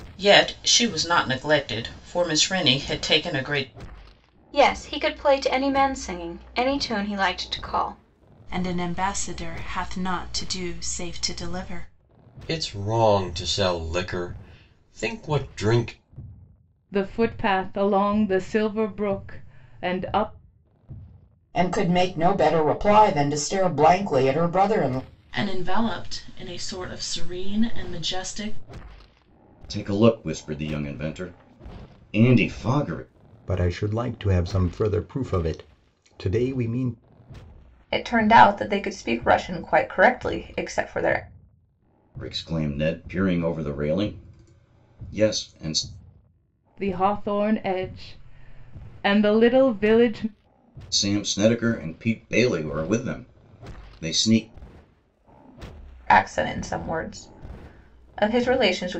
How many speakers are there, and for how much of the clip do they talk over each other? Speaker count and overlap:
ten, no overlap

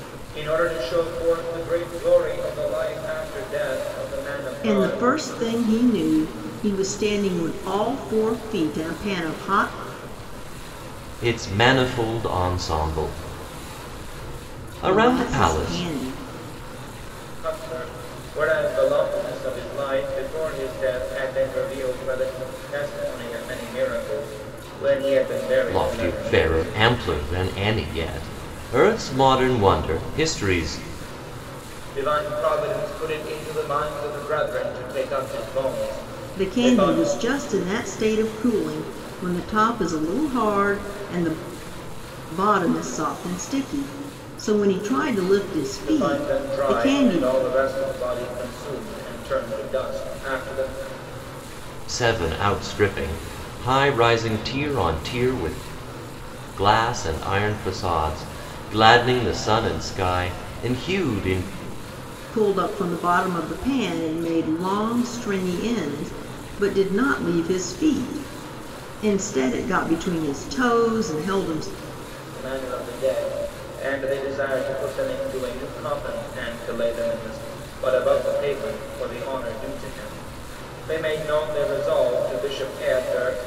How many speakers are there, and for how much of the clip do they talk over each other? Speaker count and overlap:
three, about 6%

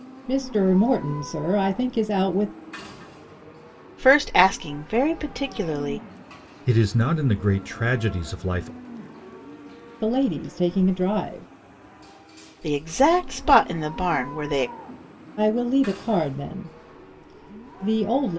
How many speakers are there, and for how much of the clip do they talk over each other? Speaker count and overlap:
three, no overlap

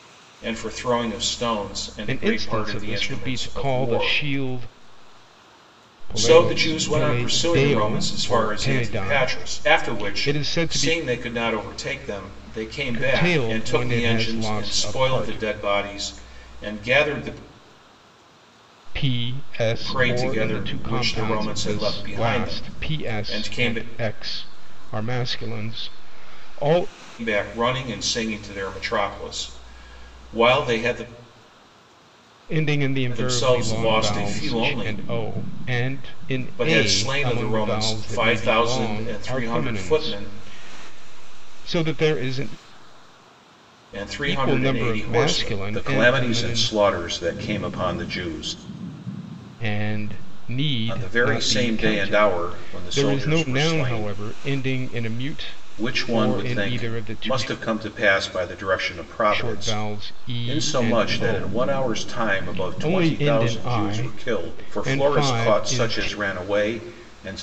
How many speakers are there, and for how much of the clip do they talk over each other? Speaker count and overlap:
two, about 49%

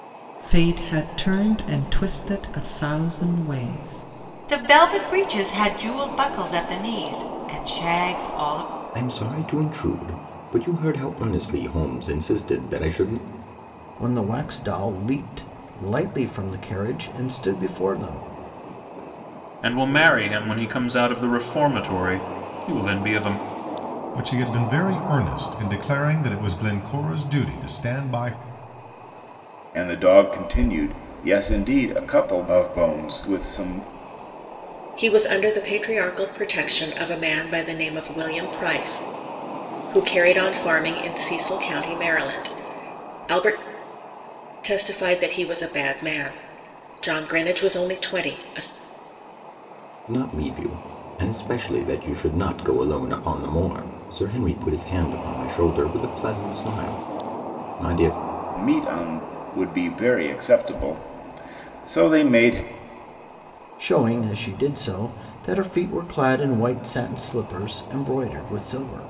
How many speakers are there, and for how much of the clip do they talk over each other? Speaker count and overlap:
eight, no overlap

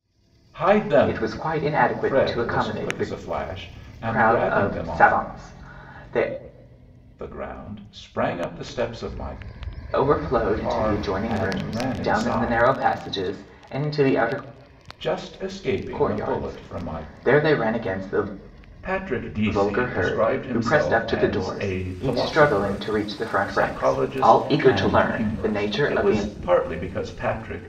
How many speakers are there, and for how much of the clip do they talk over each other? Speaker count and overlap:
two, about 46%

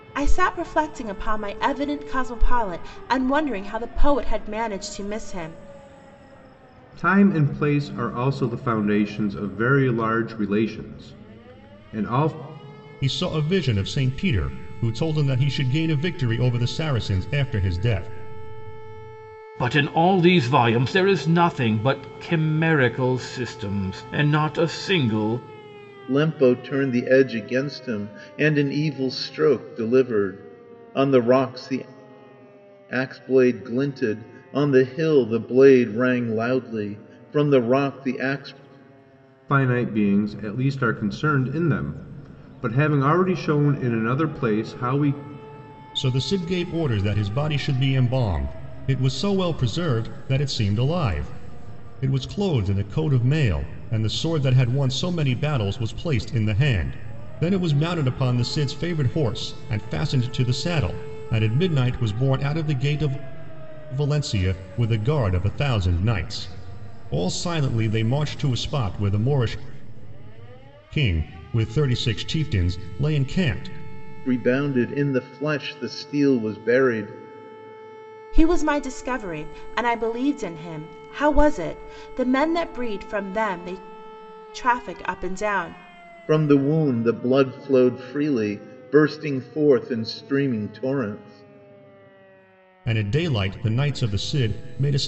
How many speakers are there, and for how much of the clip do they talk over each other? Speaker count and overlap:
five, no overlap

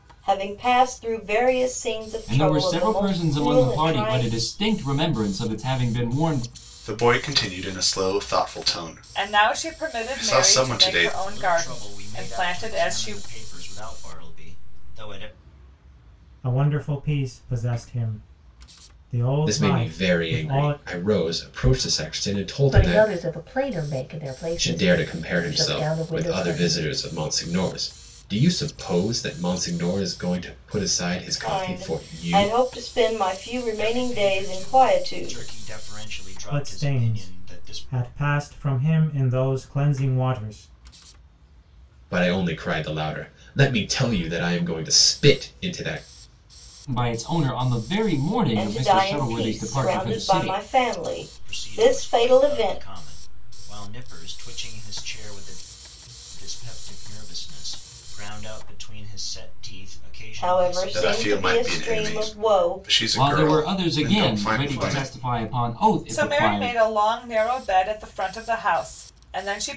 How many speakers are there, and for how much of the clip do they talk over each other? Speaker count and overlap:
eight, about 35%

